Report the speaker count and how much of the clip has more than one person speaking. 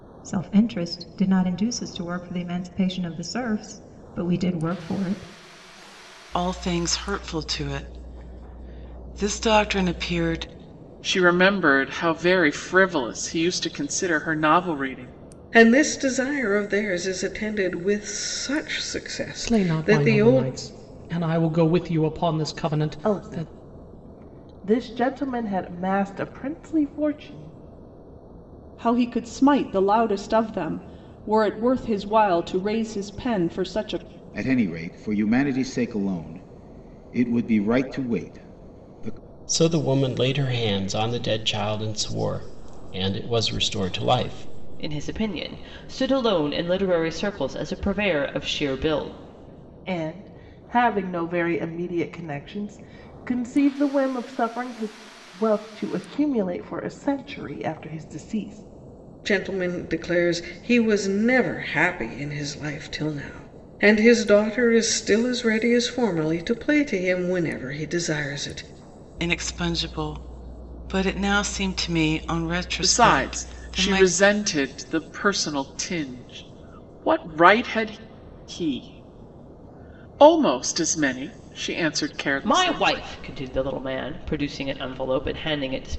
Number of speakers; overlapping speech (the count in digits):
10, about 4%